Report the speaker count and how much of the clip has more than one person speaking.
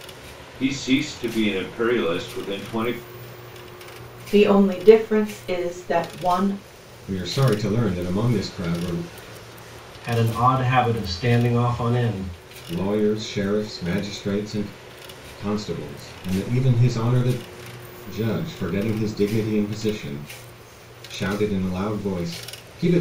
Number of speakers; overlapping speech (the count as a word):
four, no overlap